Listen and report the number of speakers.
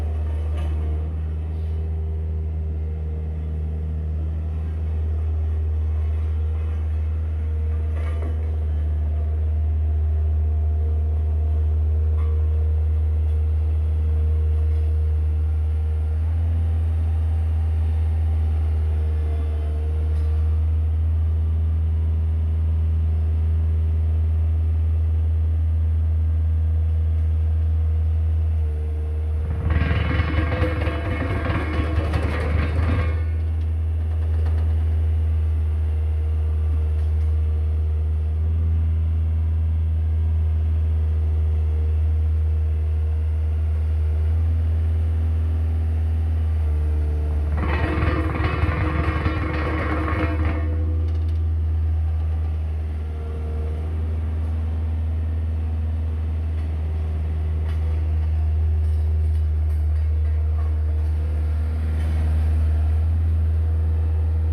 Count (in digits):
0